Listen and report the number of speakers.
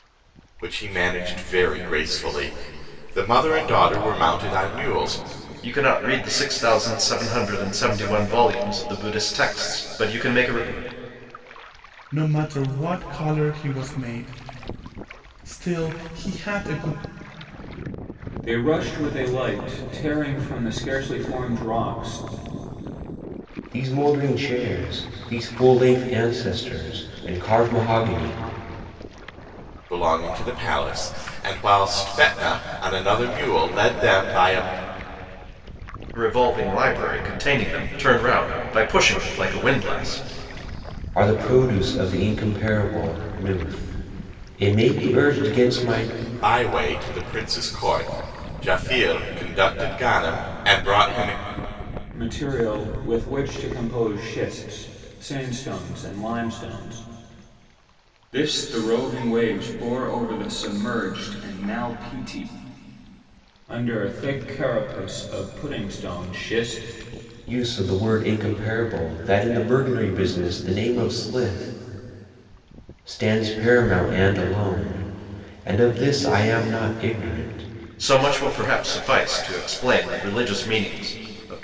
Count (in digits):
5